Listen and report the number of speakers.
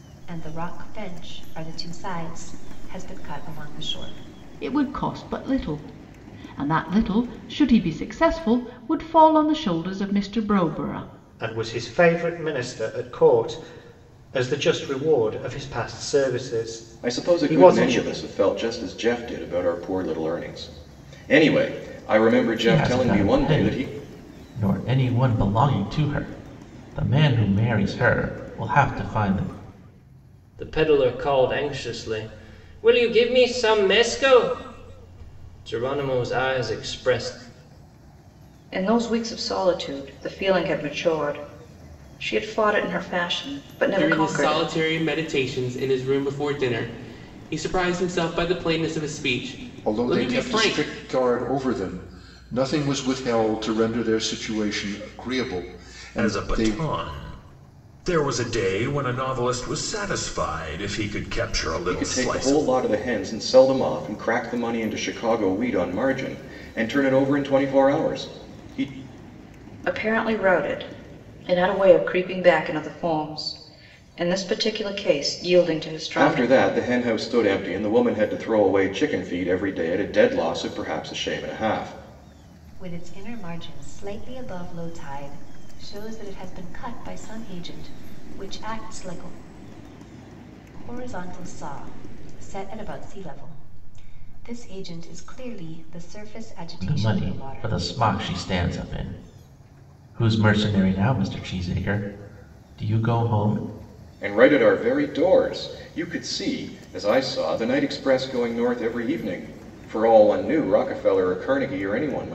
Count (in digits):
10